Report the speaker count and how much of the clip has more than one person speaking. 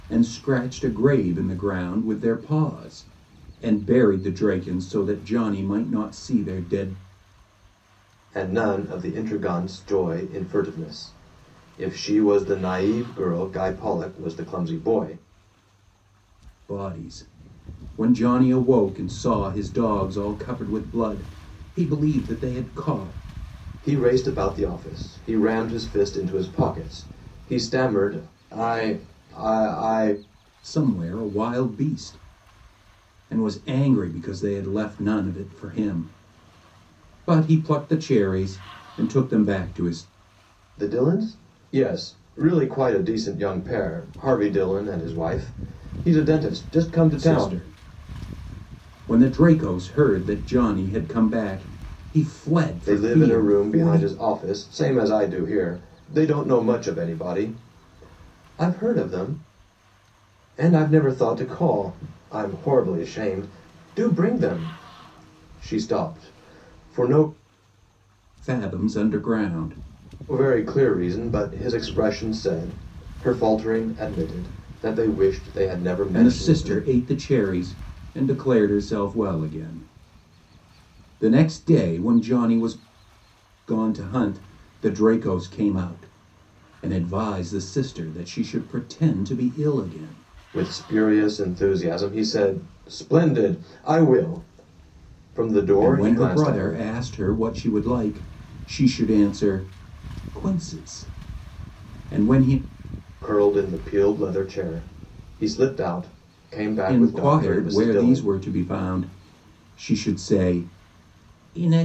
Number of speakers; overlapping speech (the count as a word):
two, about 4%